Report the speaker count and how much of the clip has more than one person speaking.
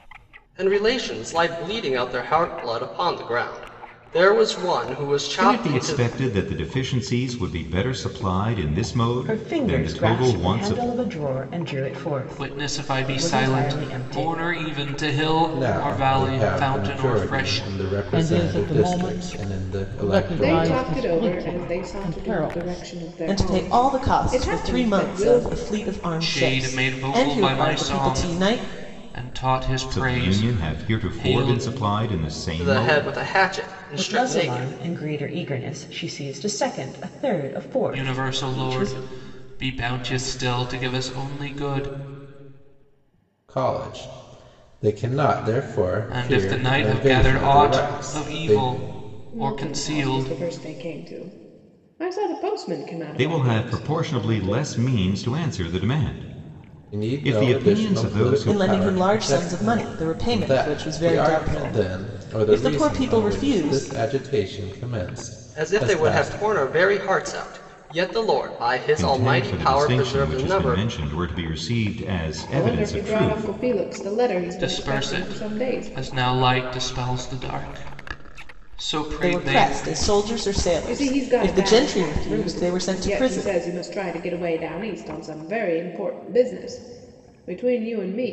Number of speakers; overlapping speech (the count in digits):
8, about 46%